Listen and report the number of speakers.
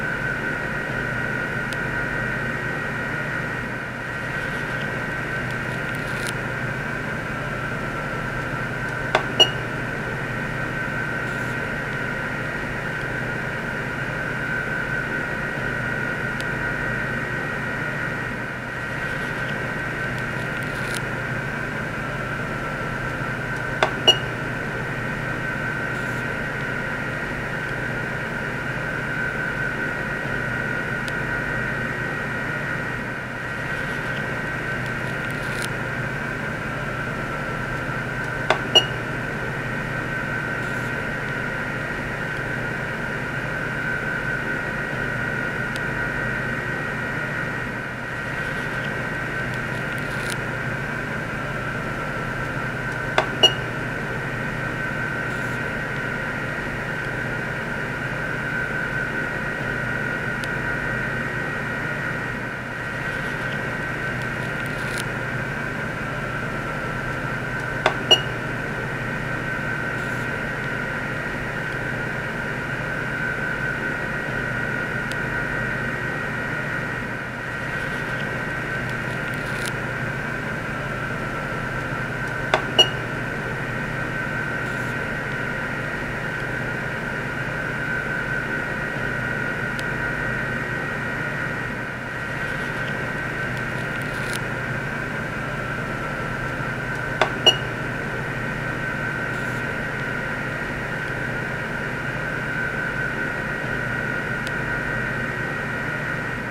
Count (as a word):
zero